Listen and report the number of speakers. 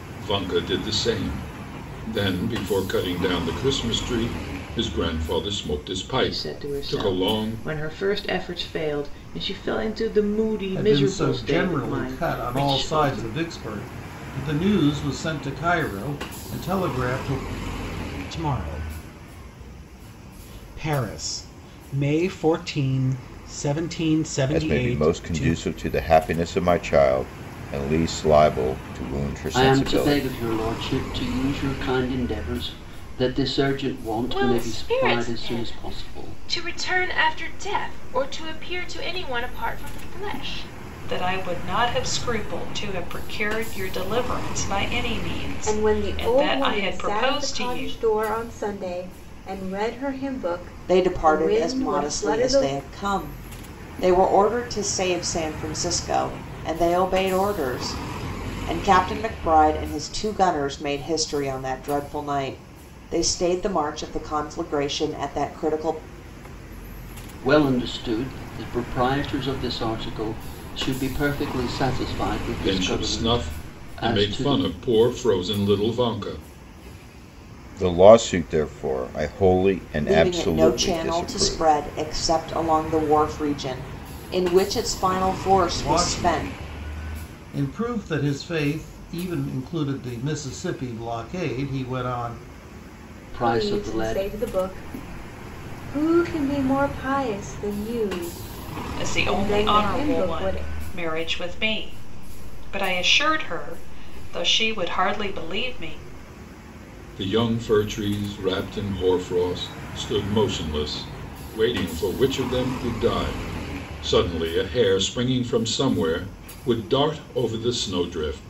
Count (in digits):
10